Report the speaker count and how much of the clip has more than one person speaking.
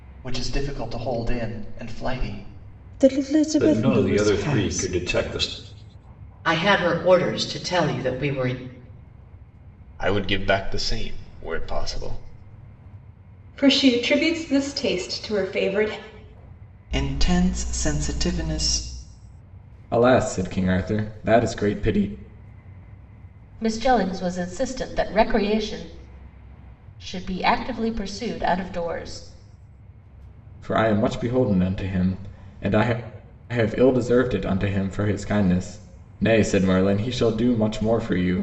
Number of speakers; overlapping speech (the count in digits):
9, about 4%